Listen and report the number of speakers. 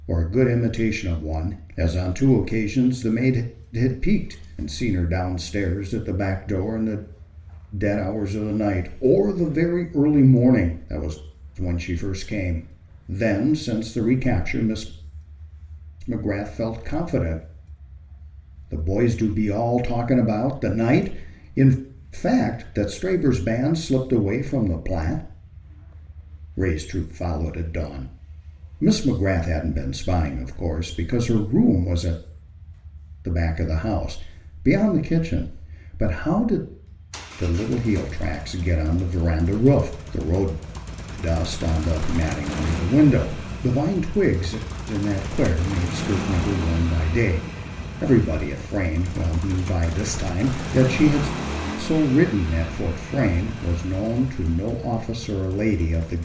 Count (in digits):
1